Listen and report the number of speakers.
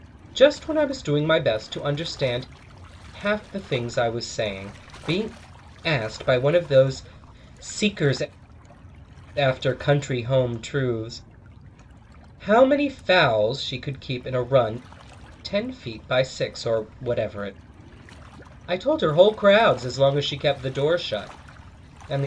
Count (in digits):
1